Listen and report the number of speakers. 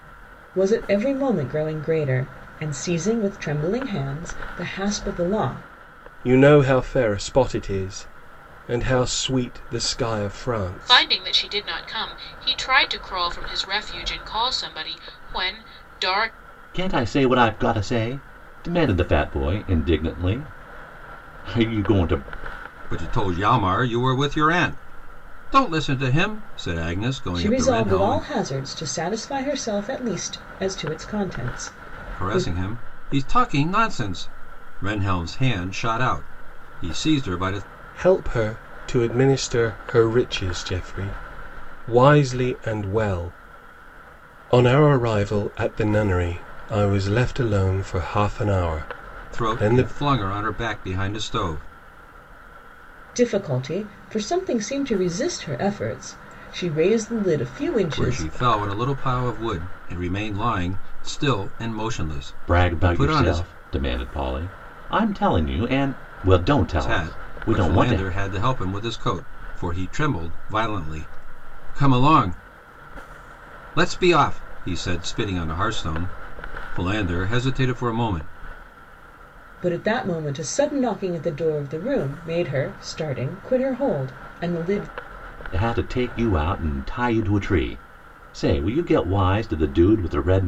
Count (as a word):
five